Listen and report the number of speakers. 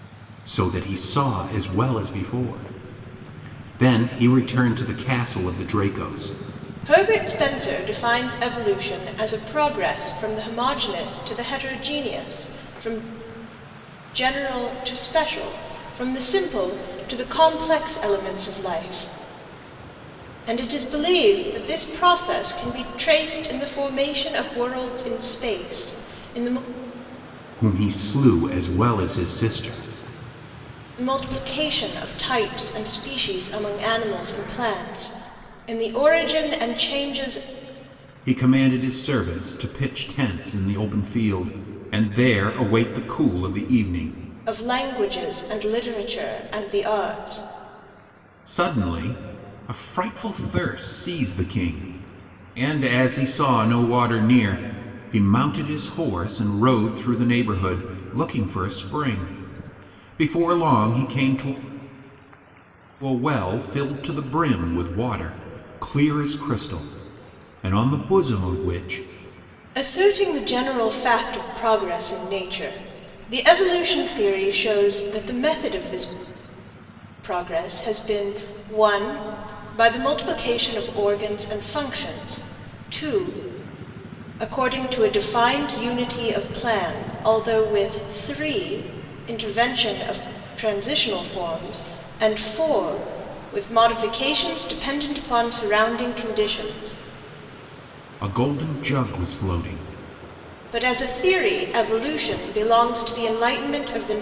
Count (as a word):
two